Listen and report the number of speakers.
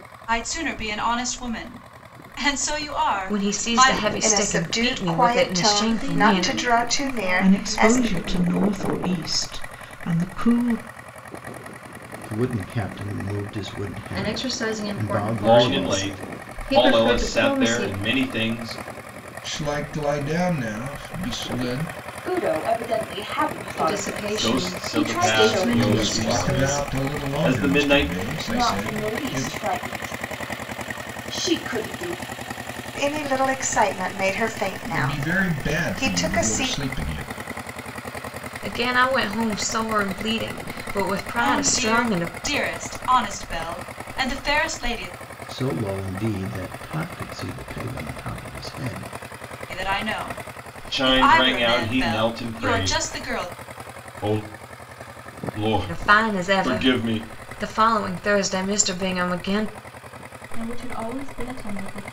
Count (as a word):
ten